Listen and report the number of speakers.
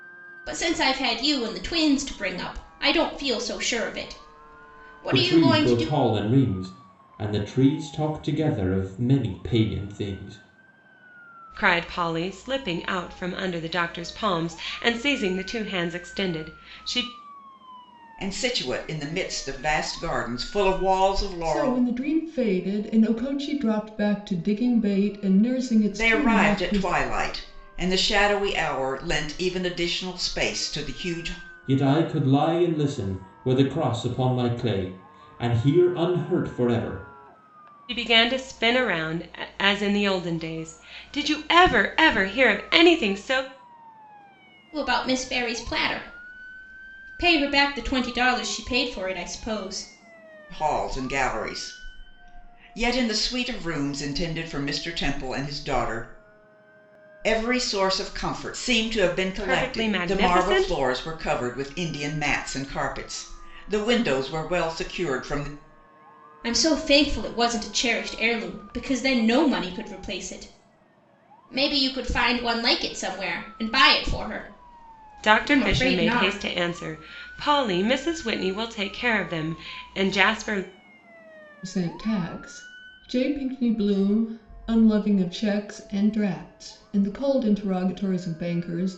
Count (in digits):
5